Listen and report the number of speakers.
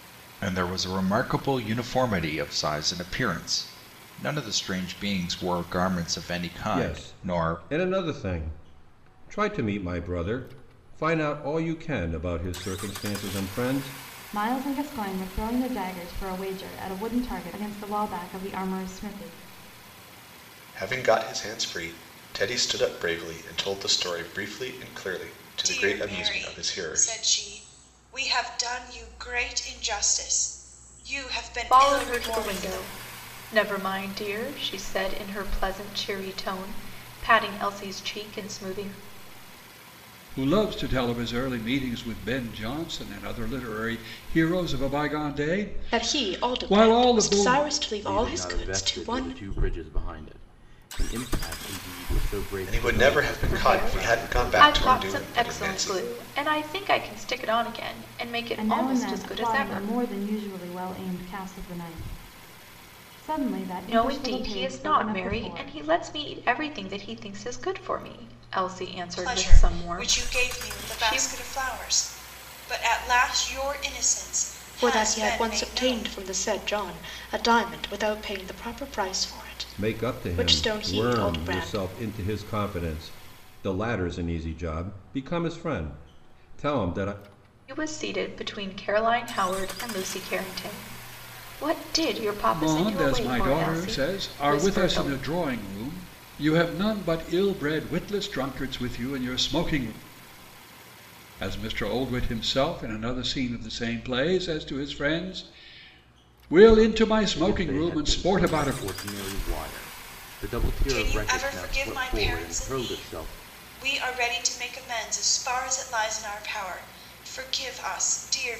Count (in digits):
9